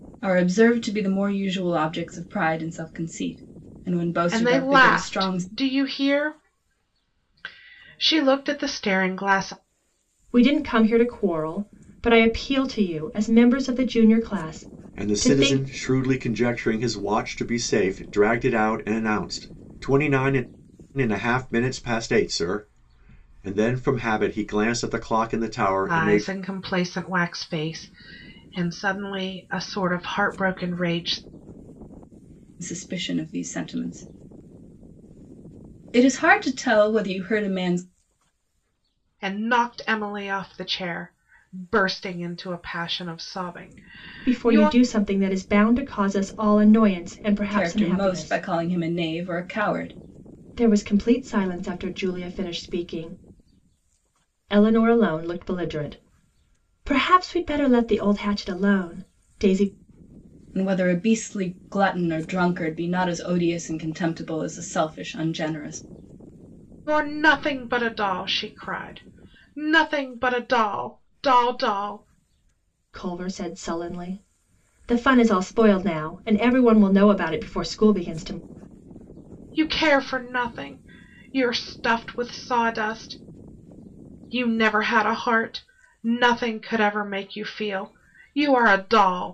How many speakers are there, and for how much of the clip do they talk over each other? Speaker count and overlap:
4, about 4%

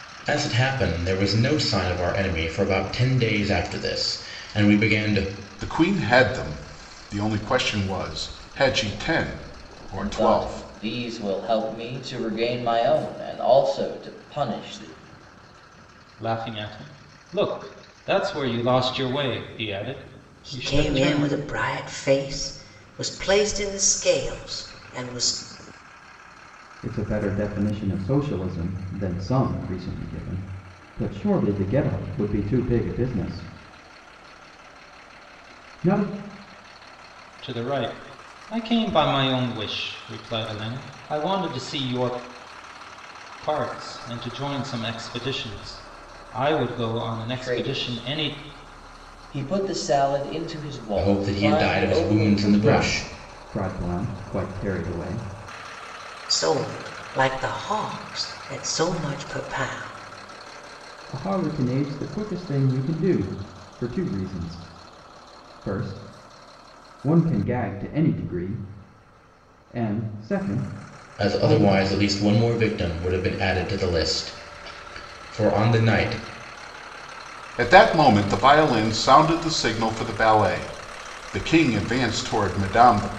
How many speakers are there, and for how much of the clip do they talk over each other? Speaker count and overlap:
6, about 6%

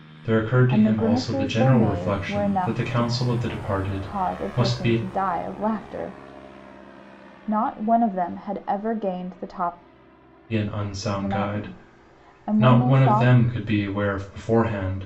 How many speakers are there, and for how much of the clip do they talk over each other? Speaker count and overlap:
2, about 38%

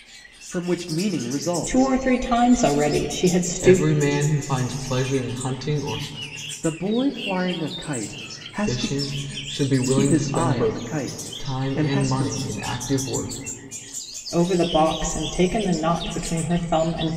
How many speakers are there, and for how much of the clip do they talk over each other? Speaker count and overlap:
3, about 18%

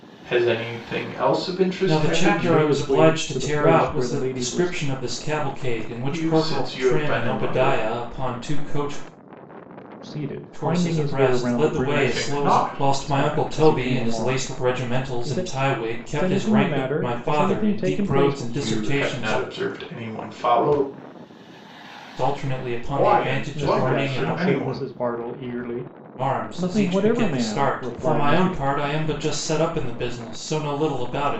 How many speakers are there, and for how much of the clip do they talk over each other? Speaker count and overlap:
3, about 53%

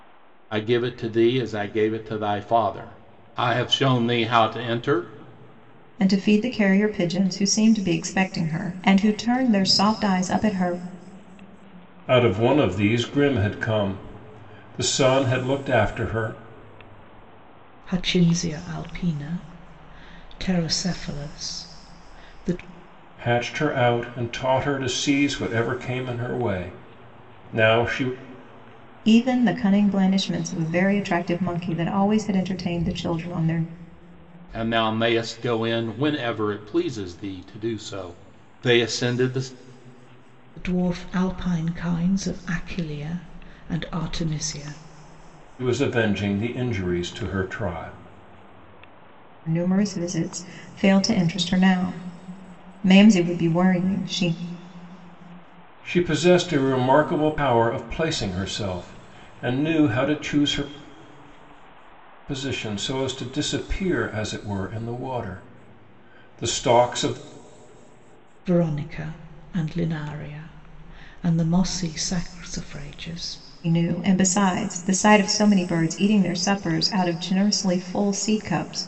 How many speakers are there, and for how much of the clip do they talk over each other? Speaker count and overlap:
4, no overlap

